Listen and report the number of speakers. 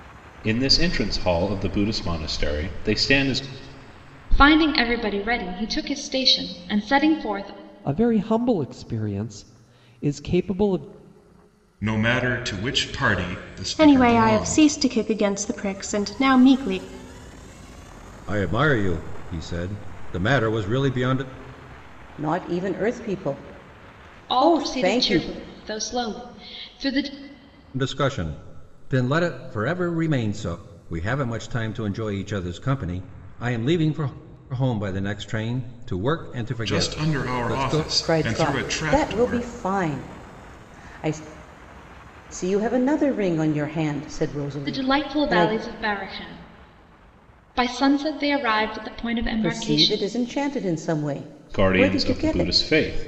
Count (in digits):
7